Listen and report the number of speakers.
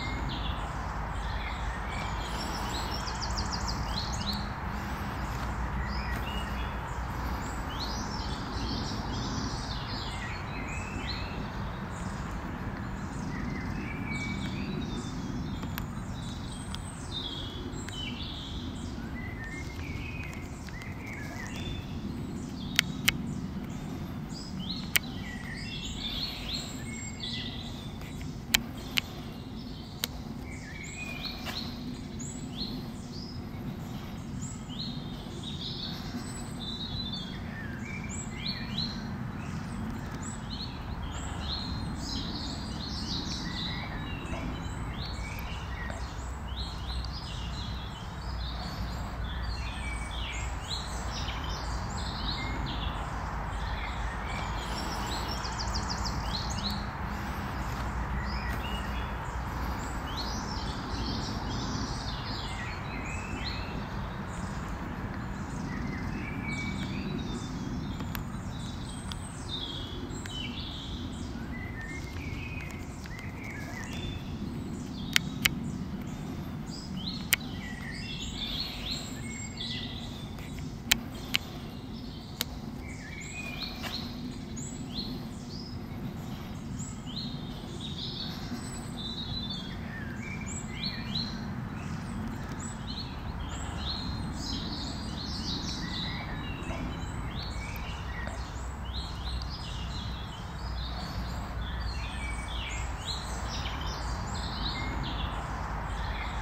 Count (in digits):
0